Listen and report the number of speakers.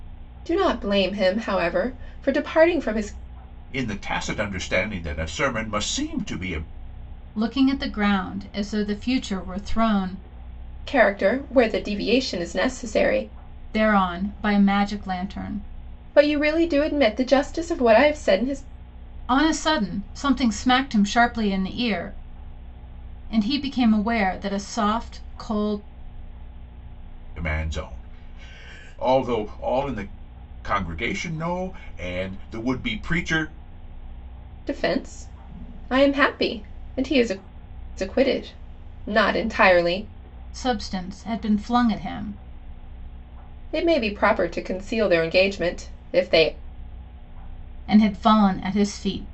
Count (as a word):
three